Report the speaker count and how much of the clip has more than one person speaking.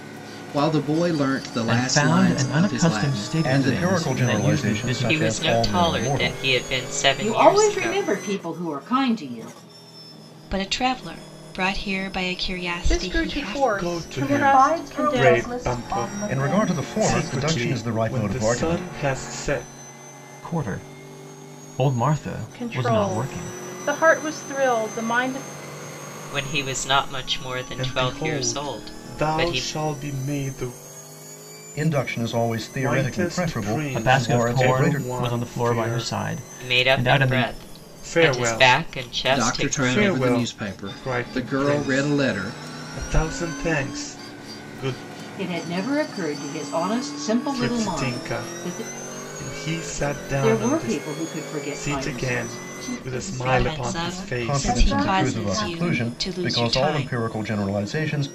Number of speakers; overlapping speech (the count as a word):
nine, about 53%